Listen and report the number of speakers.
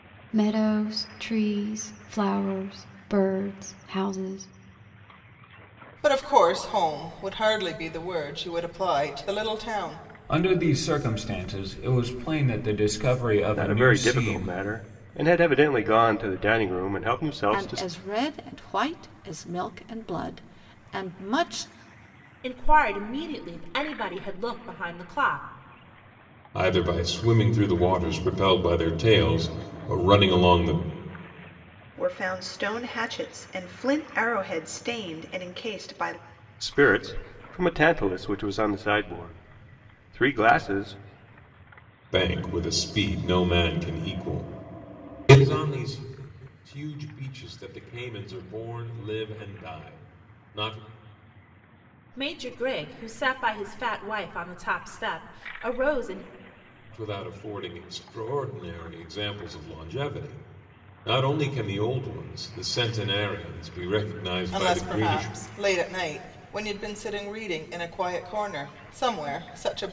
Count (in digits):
8